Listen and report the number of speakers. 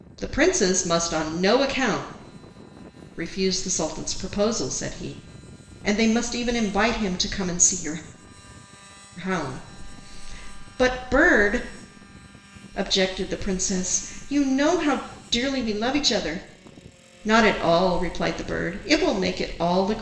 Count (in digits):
1